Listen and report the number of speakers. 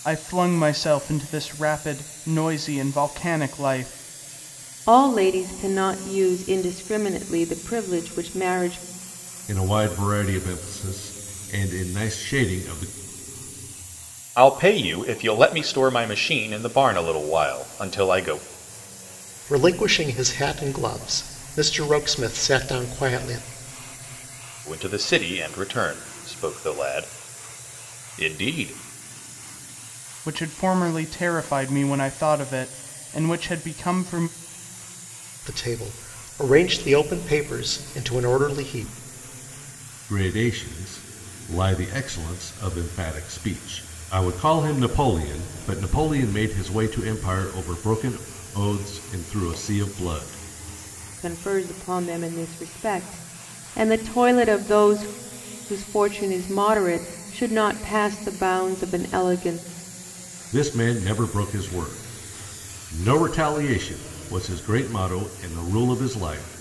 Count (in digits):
5